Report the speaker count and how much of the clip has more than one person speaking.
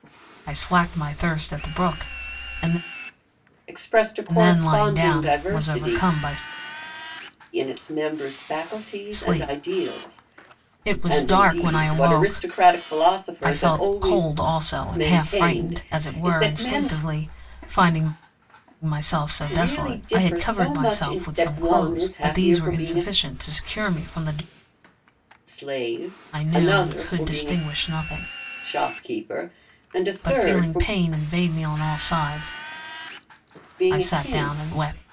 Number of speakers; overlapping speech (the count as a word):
two, about 37%